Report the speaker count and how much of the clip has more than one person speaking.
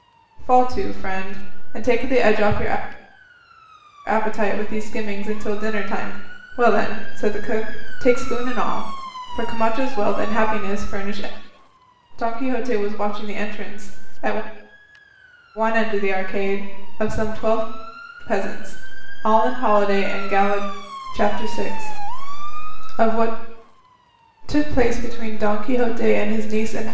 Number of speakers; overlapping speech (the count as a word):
one, no overlap